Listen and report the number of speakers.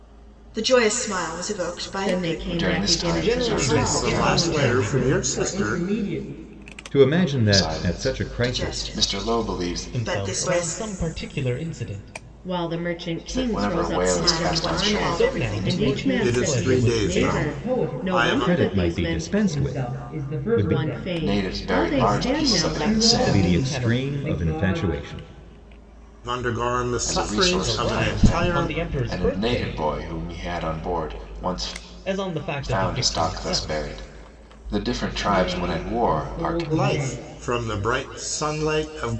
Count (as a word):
seven